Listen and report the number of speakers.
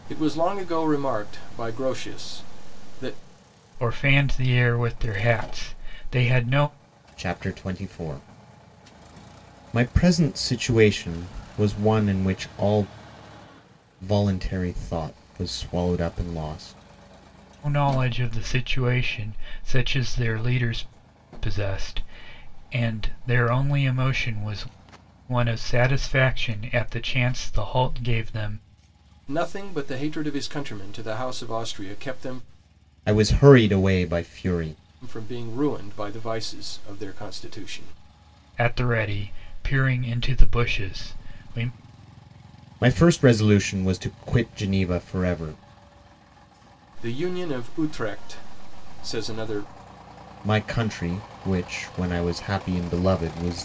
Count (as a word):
three